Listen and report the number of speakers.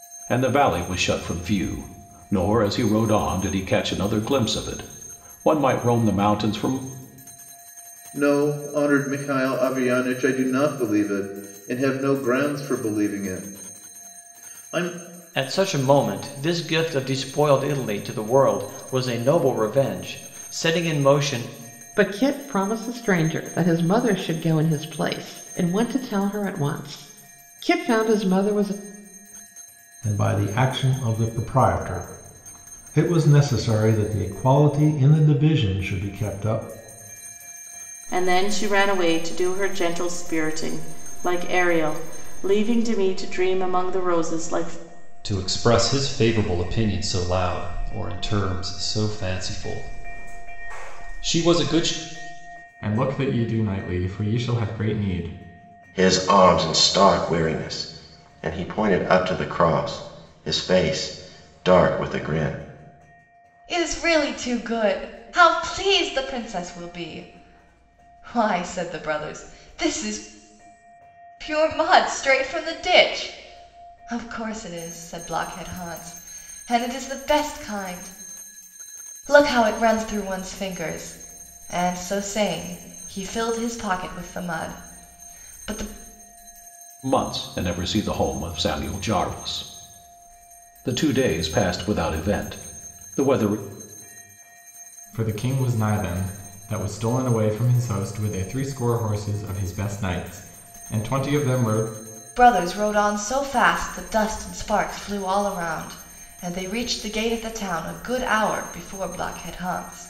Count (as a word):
ten